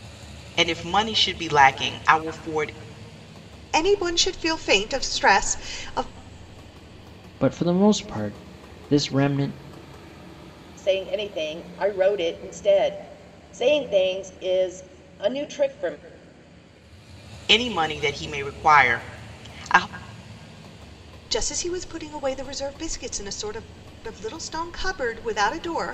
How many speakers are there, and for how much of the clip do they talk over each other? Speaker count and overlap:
four, no overlap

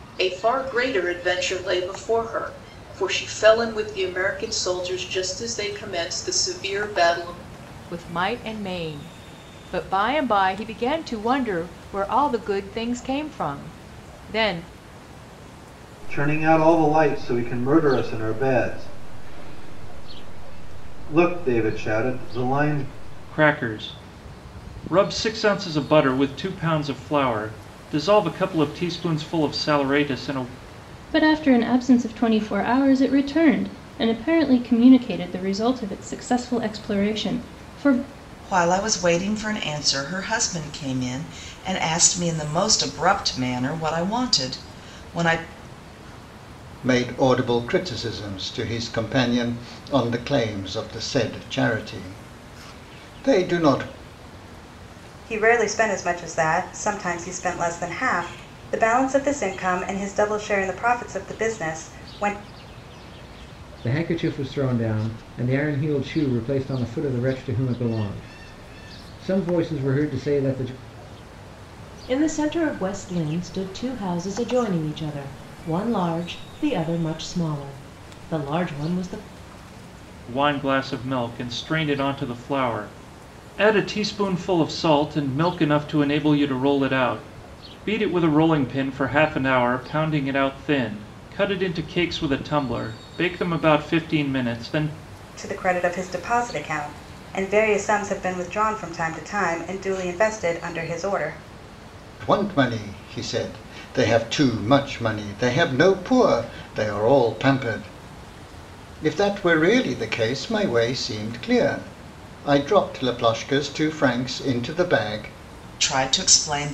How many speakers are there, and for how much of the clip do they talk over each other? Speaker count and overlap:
ten, no overlap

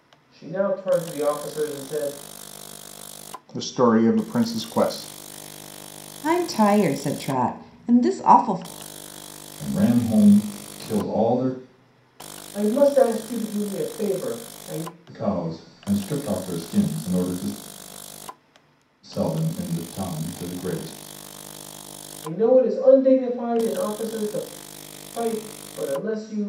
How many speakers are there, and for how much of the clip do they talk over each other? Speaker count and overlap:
four, no overlap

